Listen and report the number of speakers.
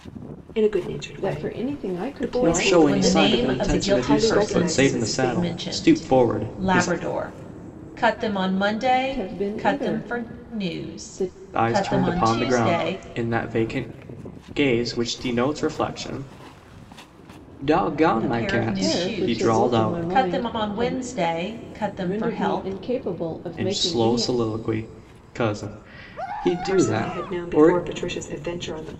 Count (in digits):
4